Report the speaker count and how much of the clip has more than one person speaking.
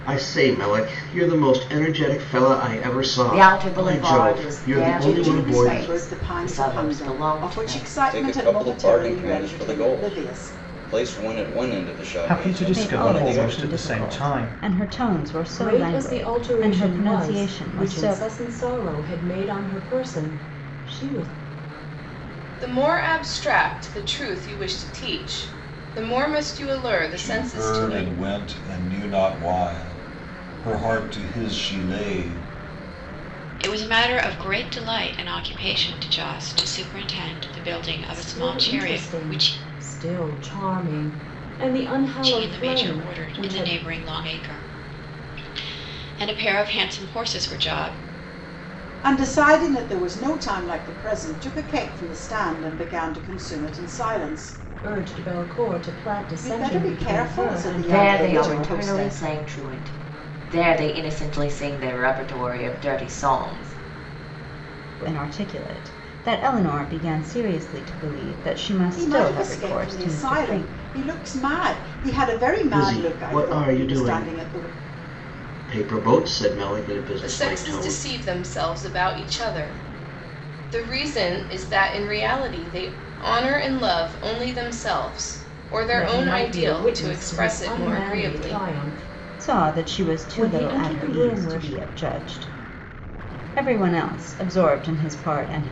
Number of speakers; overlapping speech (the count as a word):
ten, about 30%